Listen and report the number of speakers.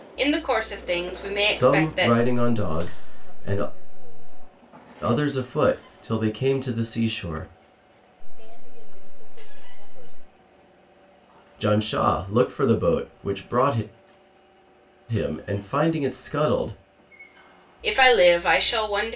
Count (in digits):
3